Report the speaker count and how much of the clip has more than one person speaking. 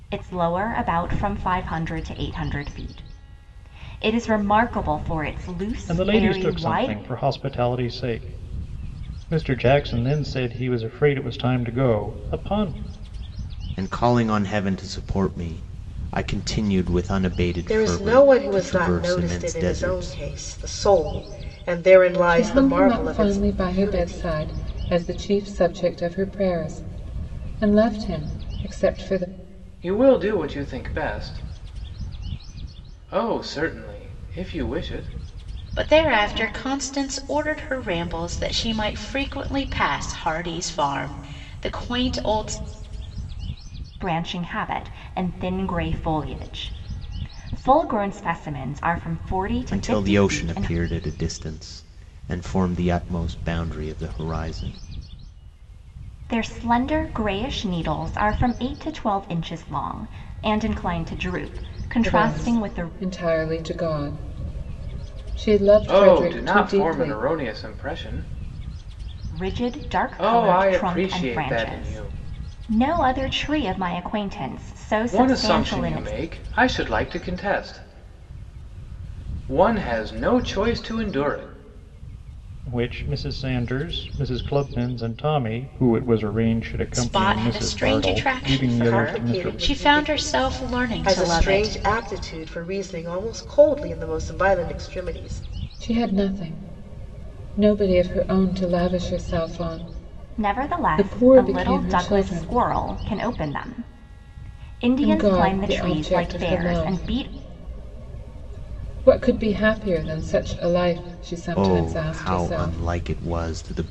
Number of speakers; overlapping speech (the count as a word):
seven, about 21%